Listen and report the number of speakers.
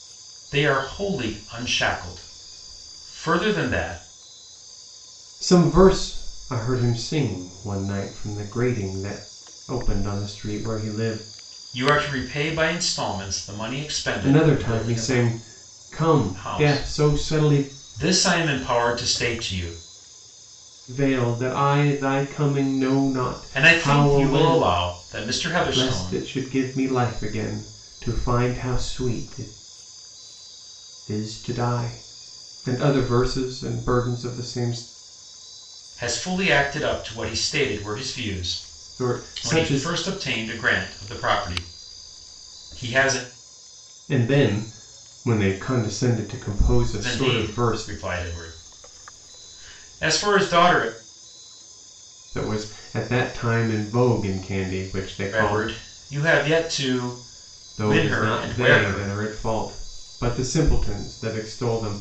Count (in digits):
2